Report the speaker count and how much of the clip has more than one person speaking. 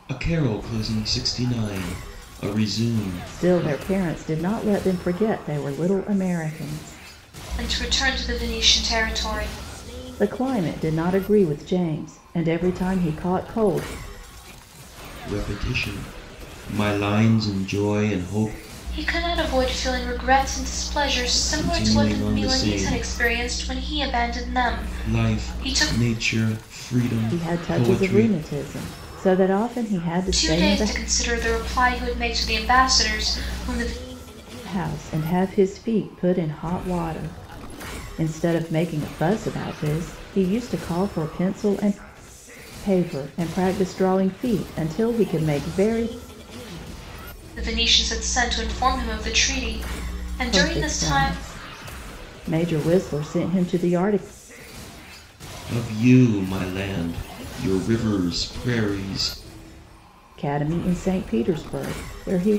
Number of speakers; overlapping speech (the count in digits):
3, about 9%